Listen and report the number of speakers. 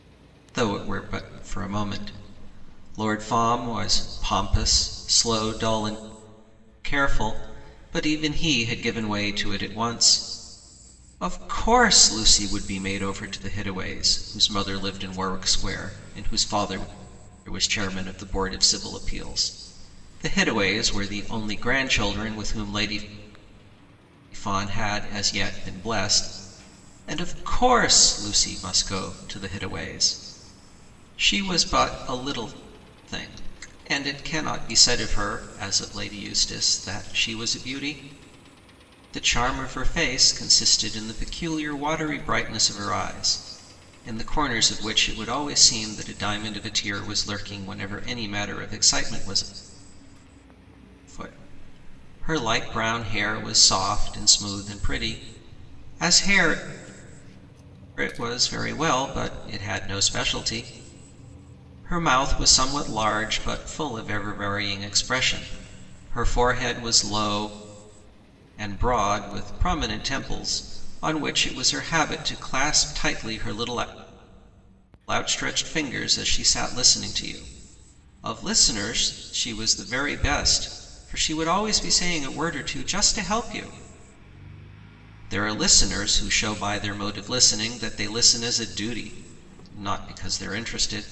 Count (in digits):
1